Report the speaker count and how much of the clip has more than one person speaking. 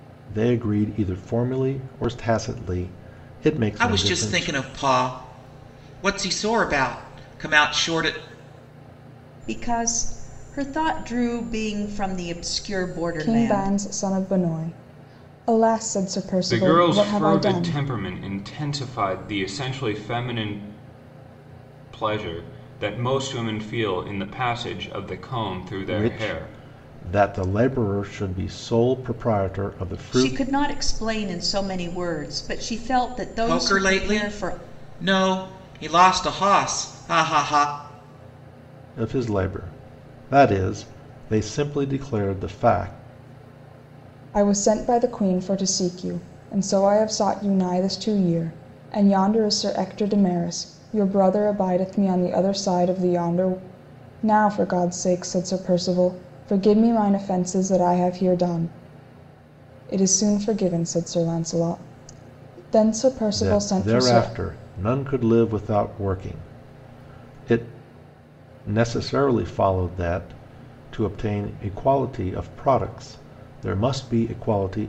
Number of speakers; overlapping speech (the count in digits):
5, about 8%